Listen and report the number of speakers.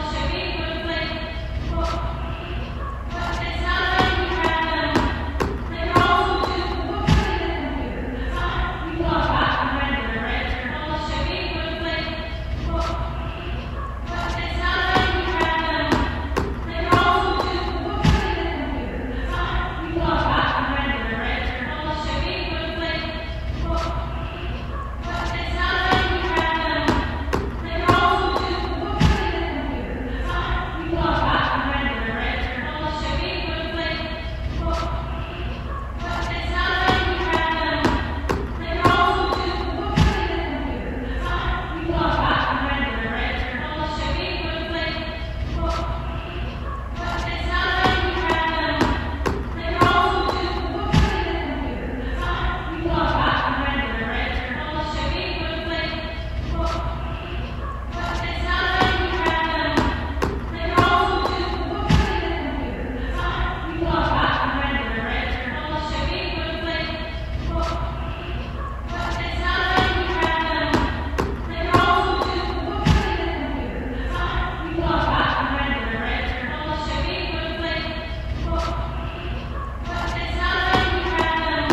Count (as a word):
zero